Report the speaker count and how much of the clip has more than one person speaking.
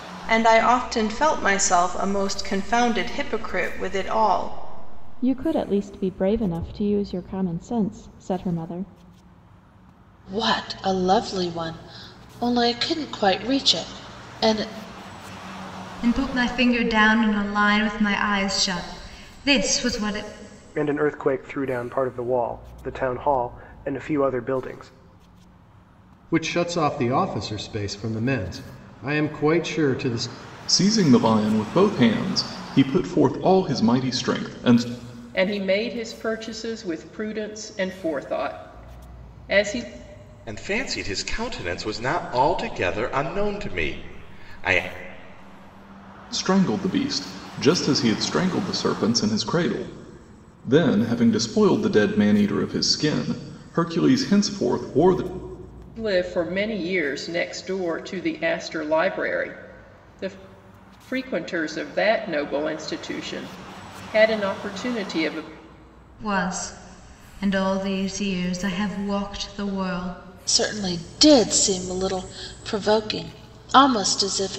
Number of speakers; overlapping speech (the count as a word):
nine, no overlap